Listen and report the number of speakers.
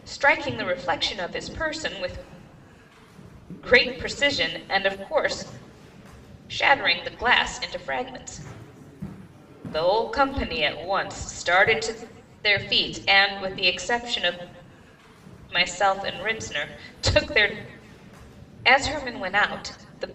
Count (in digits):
1